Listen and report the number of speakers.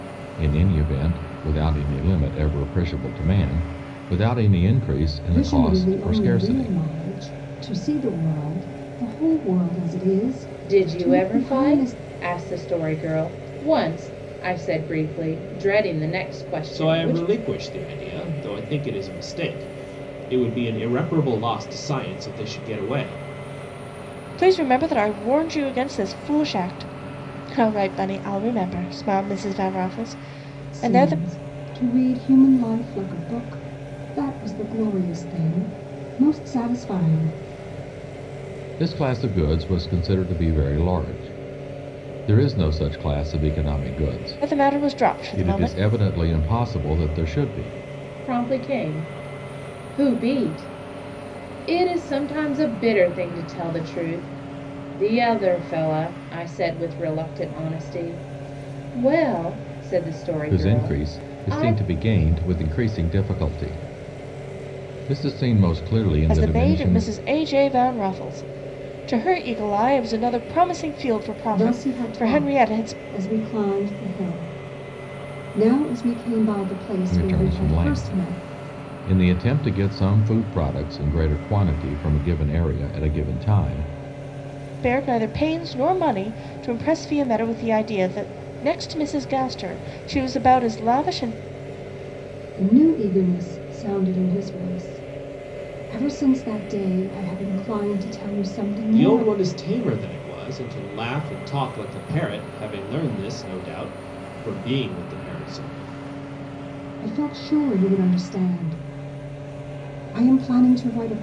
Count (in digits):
5